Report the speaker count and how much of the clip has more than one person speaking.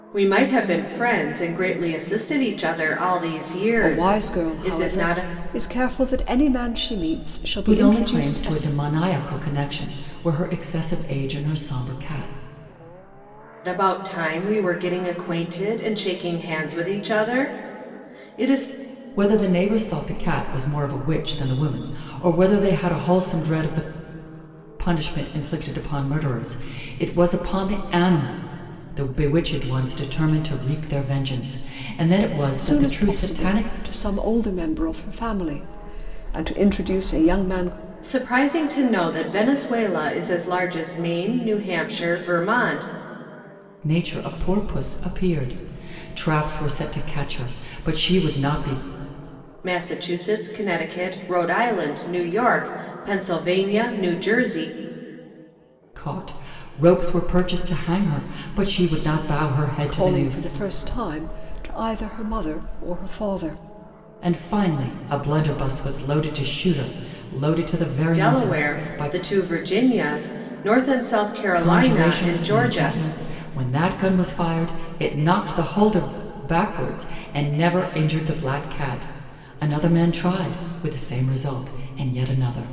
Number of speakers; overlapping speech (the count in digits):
3, about 8%